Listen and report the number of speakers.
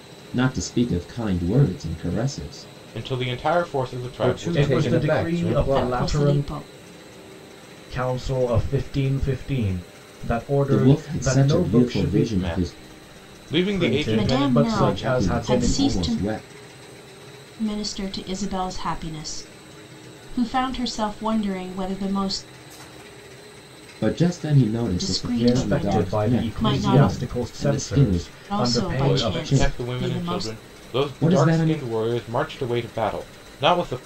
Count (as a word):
five